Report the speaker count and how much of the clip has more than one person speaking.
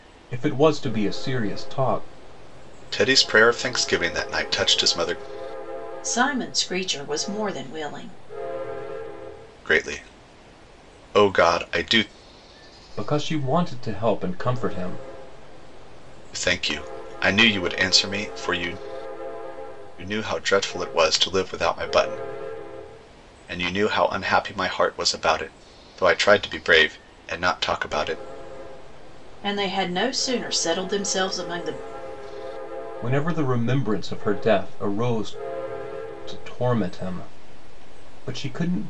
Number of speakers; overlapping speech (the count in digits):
3, no overlap